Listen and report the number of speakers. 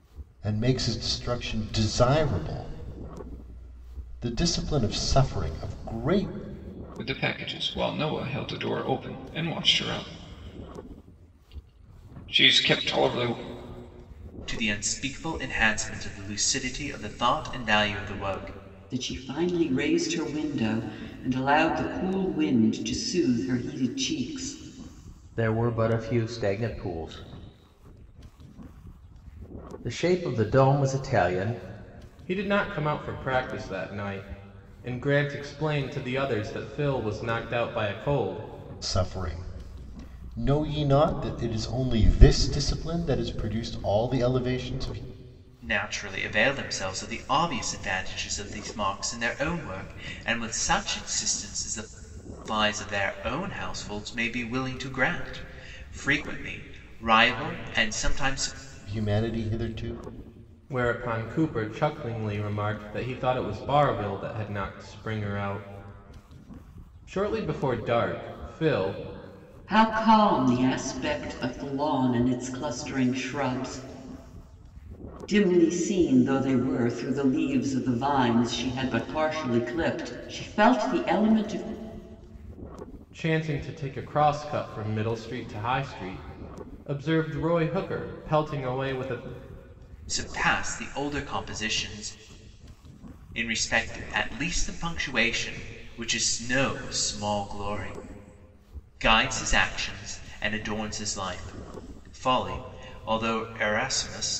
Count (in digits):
6